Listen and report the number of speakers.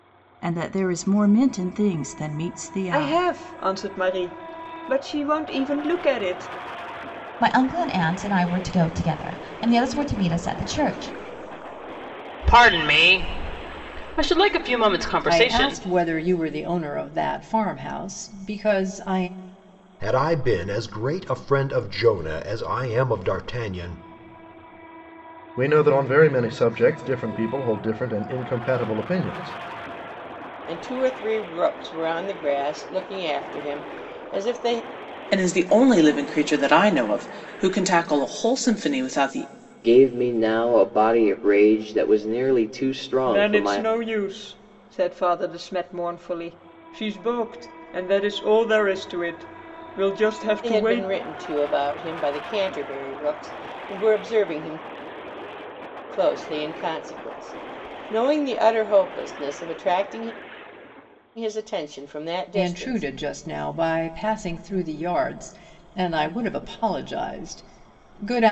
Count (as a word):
ten